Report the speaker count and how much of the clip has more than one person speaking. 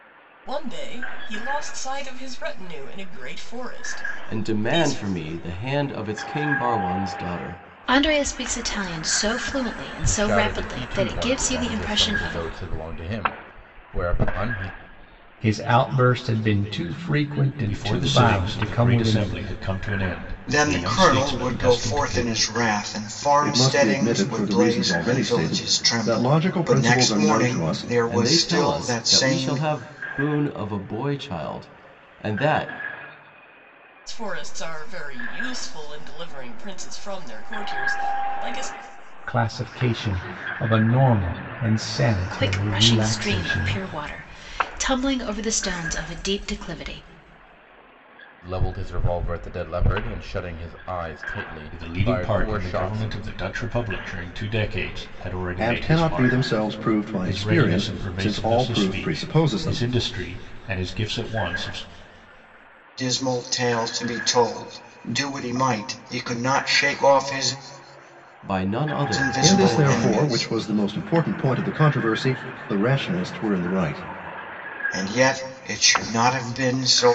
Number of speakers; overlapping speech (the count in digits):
8, about 27%